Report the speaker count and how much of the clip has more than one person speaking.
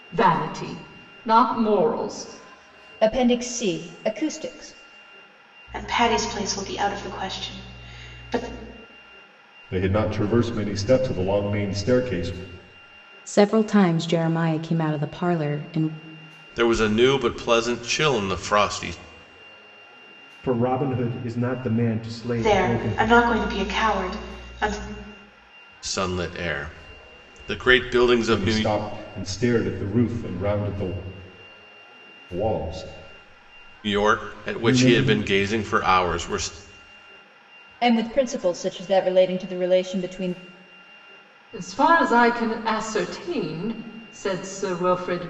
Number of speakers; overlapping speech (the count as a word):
seven, about 5%